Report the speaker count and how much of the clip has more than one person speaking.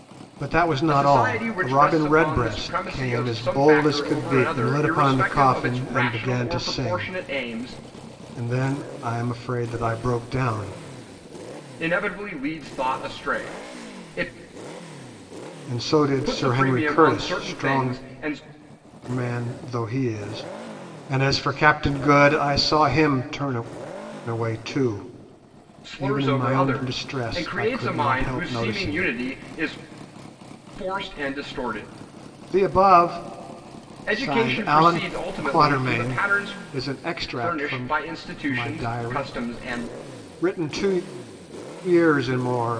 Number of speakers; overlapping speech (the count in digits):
2, about 36%